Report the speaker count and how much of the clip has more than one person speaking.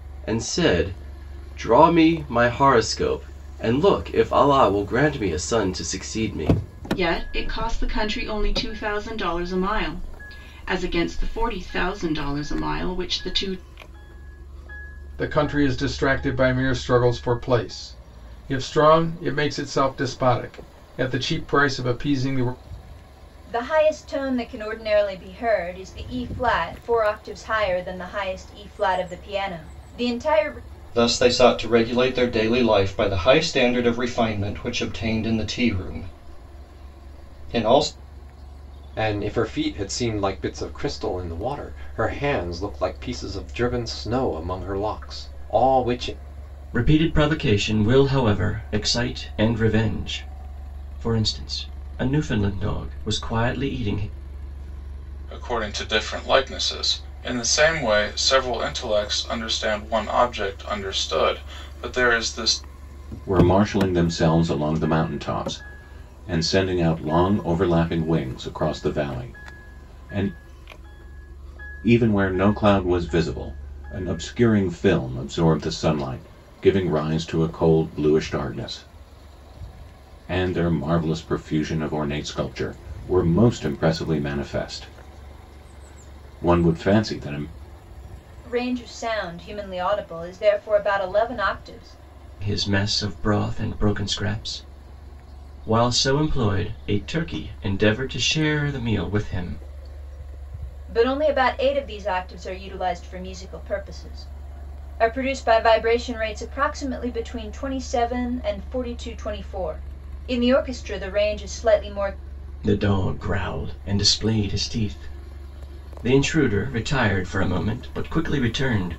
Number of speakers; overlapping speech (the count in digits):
9, no overlap